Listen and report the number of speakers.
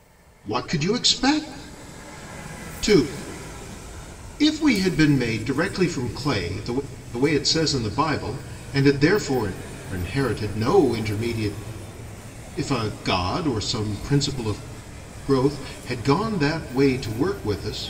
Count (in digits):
1